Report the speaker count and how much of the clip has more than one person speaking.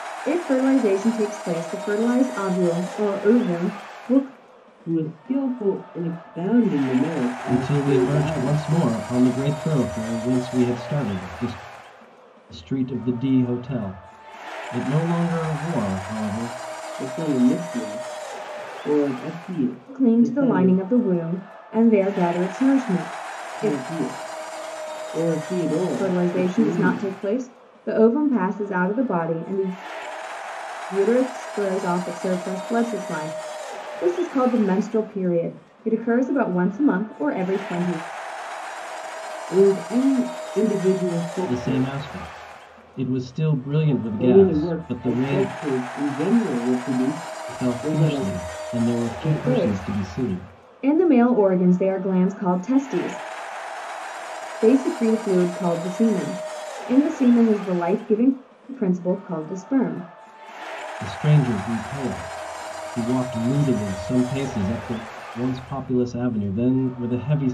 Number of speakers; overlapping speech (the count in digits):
3, about 11%